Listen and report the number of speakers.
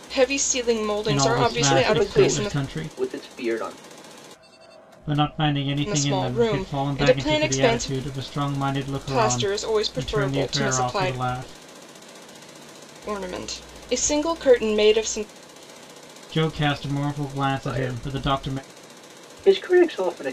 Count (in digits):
3